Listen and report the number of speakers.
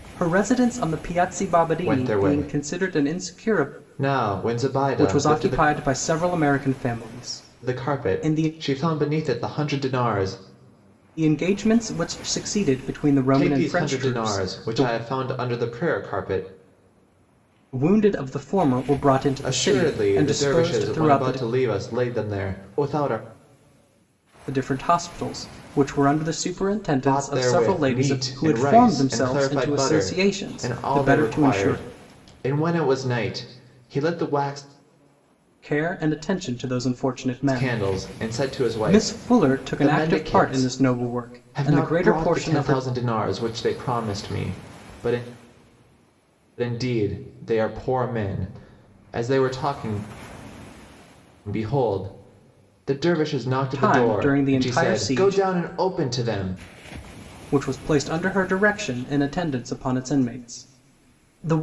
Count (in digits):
2